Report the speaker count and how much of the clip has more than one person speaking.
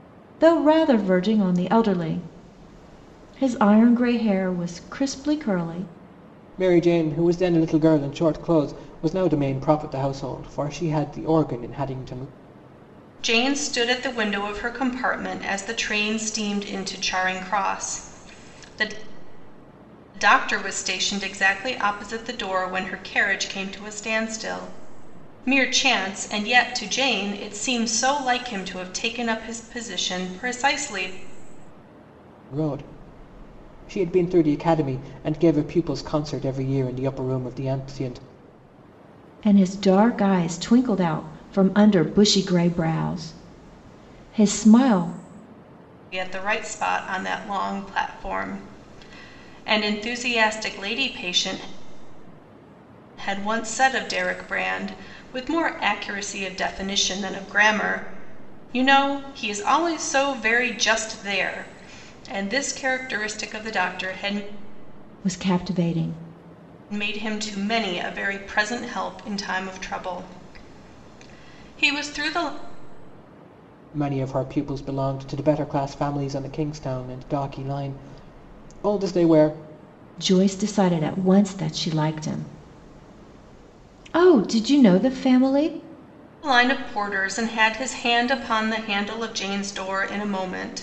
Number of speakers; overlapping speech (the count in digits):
3, no overlap